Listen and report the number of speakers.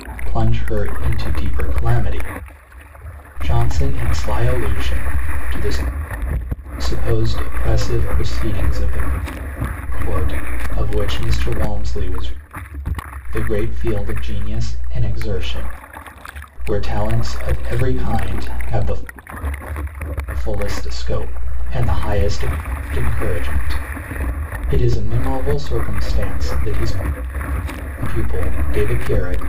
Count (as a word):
one